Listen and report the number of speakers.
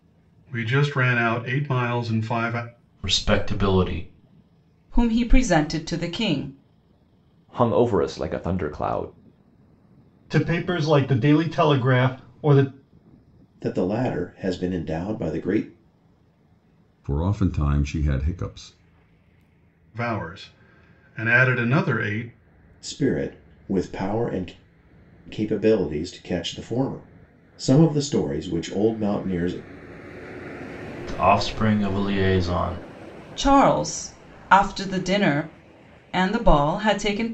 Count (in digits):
7